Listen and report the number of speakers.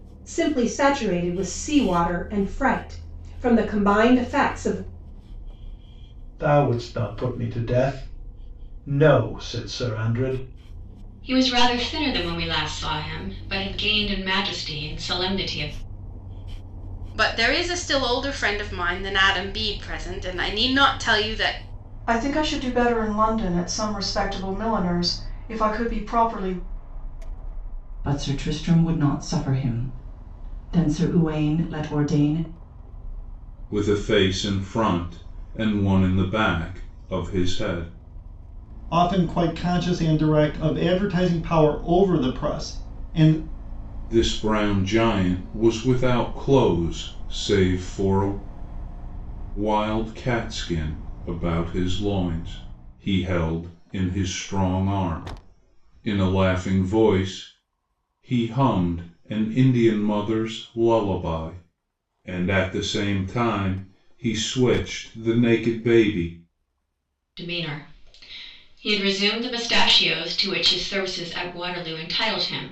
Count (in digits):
8